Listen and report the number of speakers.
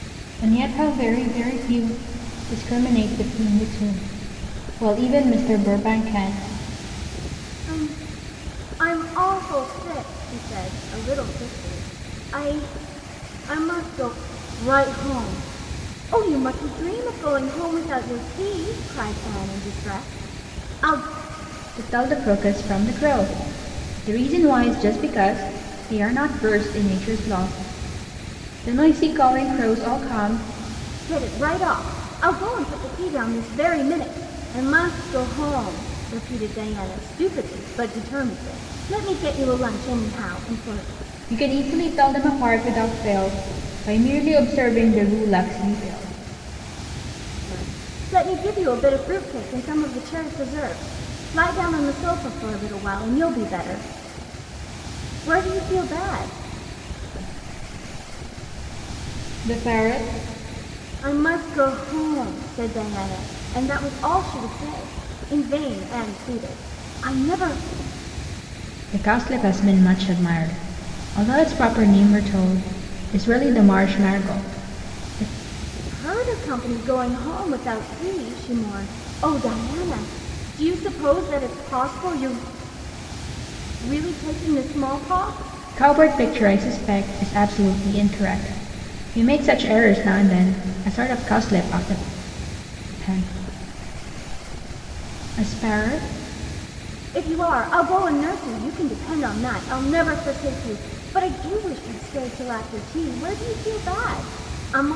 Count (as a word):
two